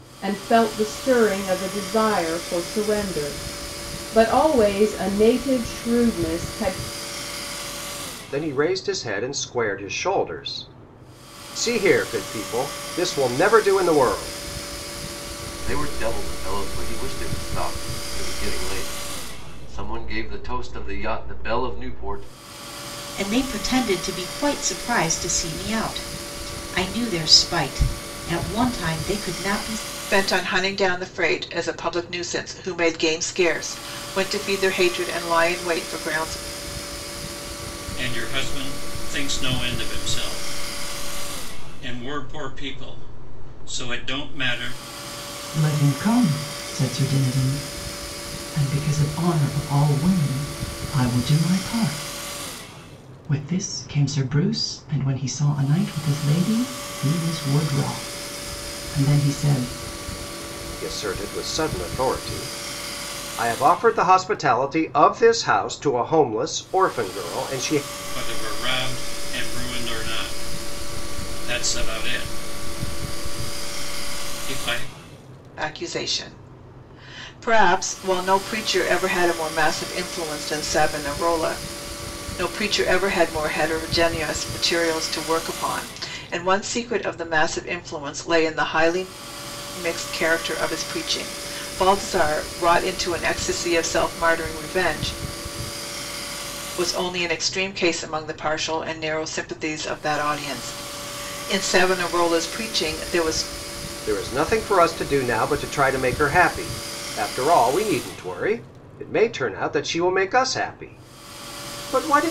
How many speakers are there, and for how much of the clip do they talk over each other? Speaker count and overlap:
7, no overlap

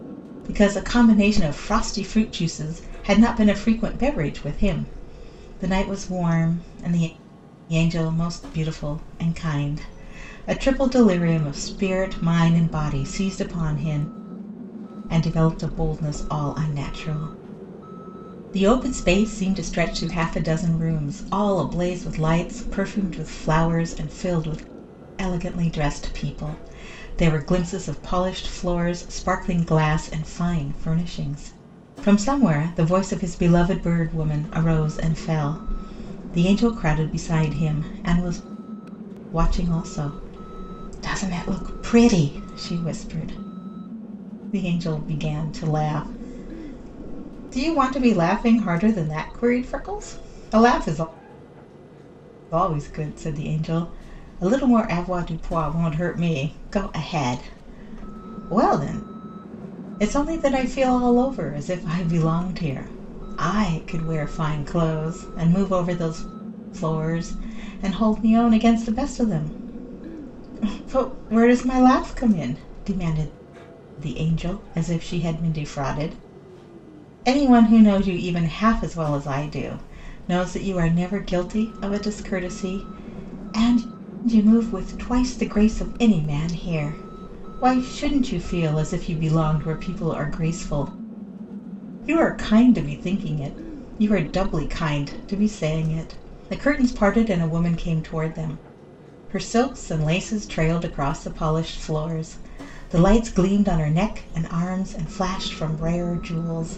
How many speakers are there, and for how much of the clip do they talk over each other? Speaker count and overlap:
1, no overlap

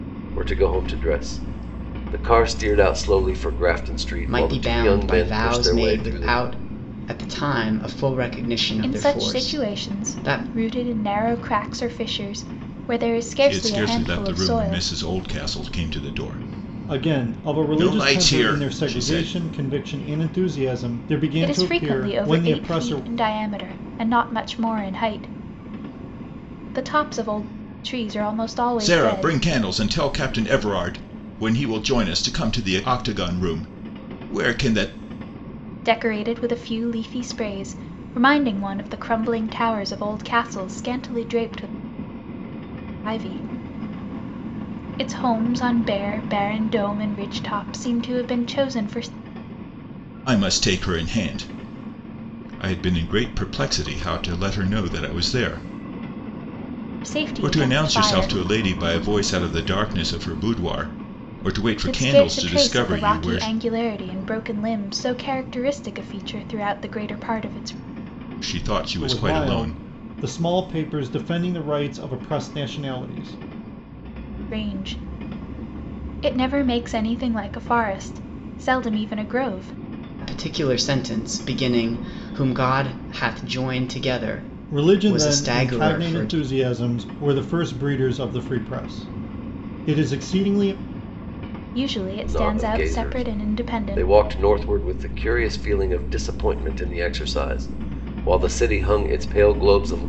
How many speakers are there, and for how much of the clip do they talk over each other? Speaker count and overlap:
5, about 17%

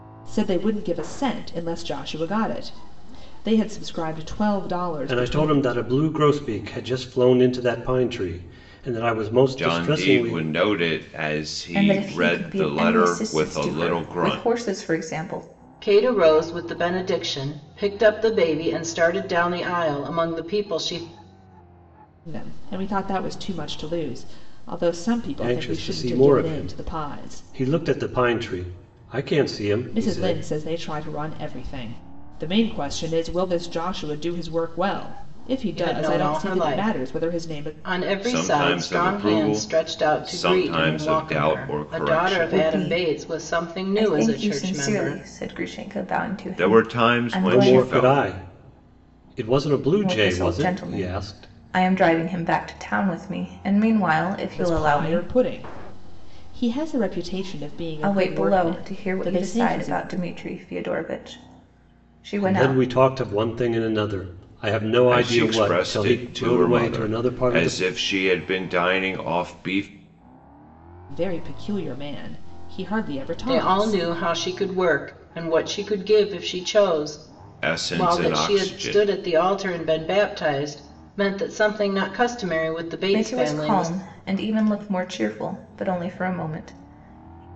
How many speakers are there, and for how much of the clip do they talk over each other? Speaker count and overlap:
5, about 32%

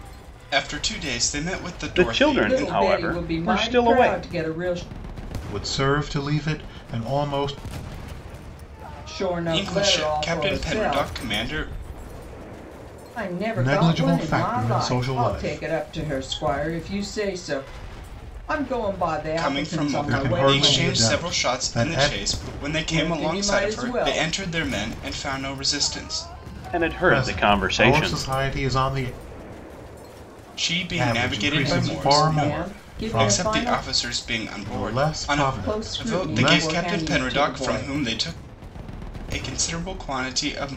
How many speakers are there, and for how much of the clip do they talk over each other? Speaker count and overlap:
4, about 44%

